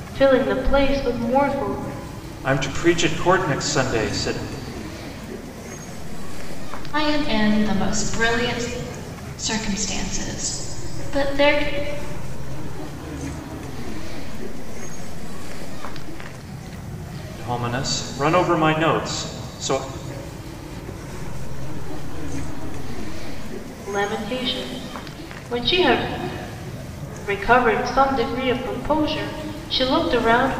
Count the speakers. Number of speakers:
four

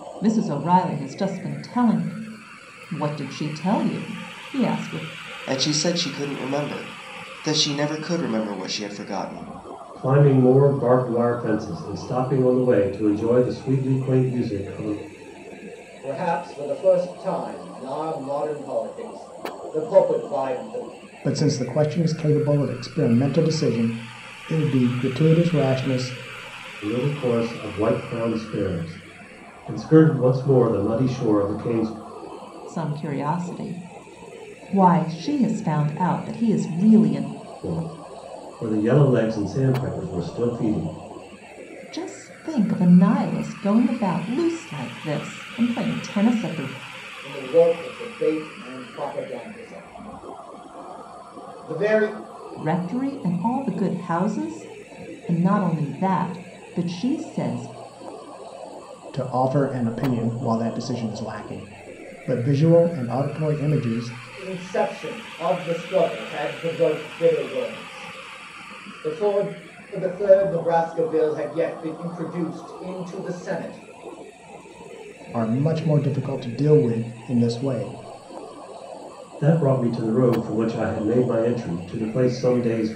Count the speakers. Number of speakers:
five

